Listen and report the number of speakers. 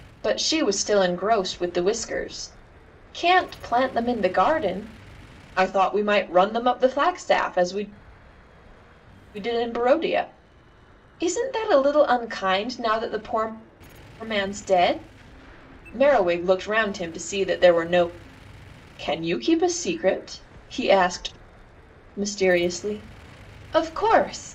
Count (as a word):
one